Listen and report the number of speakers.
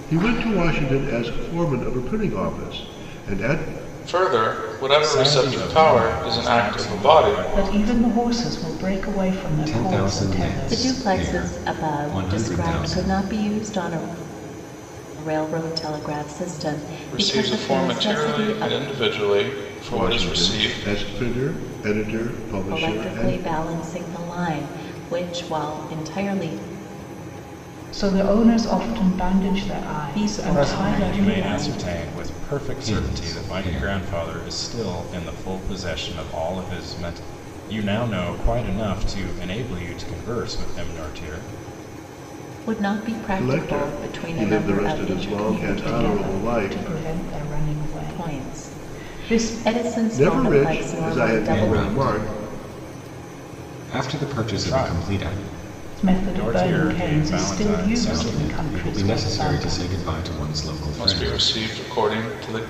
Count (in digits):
6